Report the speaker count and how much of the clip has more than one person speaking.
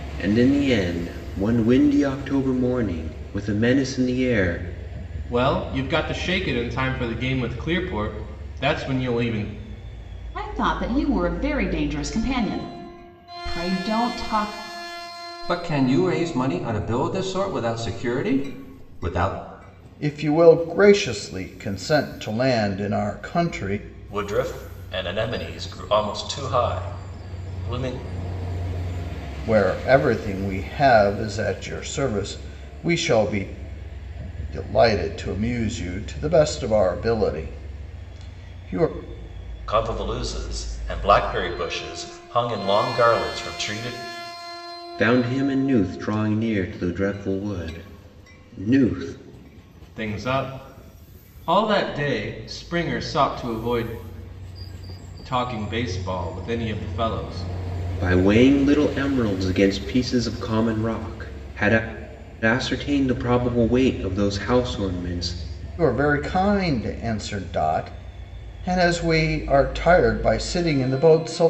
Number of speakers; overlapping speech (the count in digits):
6, no overlap